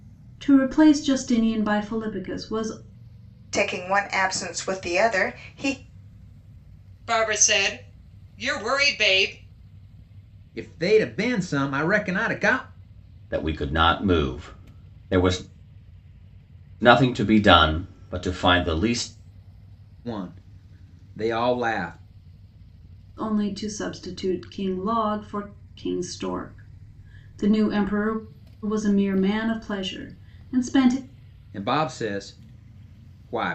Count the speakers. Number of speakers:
5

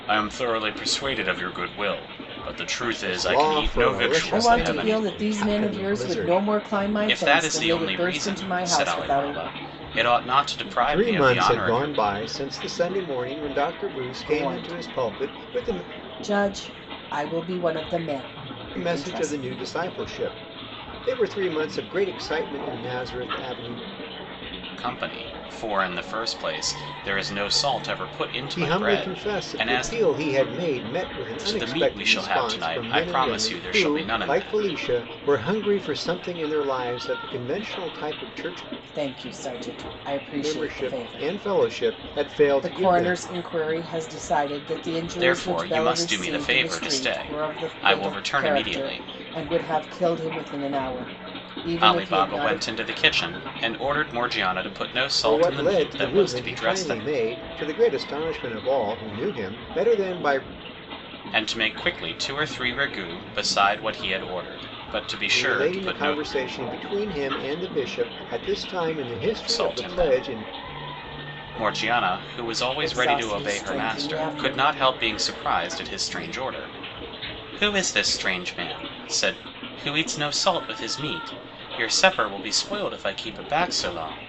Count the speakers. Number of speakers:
3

